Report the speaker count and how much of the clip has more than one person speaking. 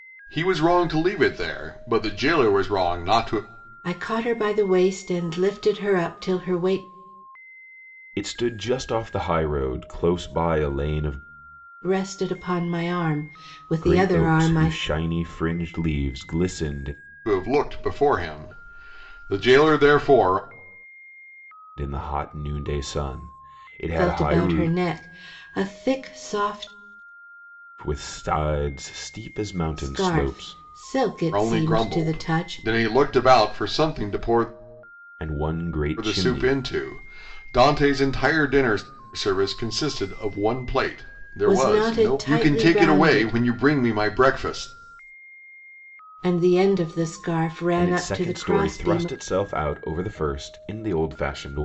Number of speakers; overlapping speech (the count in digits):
3, about 16%